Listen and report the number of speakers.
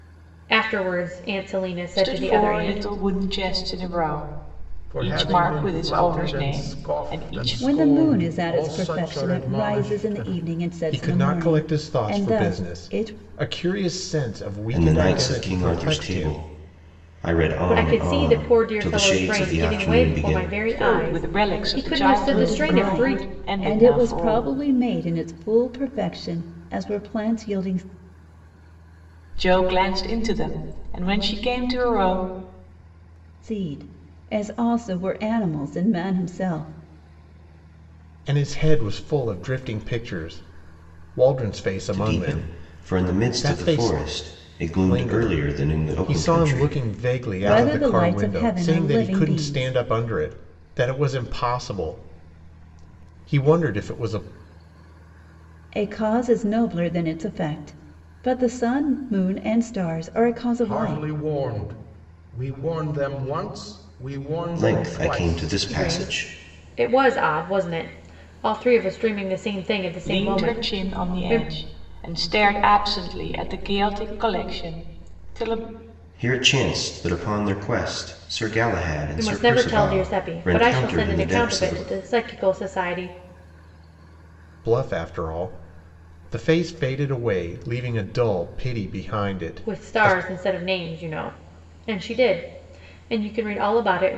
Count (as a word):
six